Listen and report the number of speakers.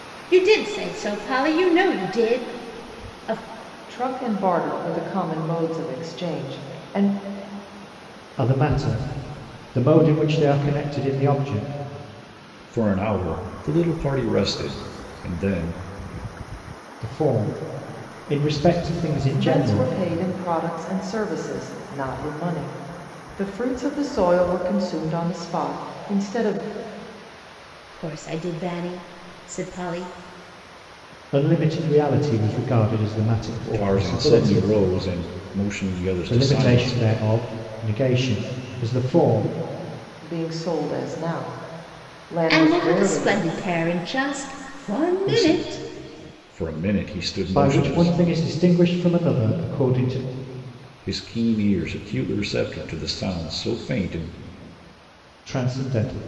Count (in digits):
4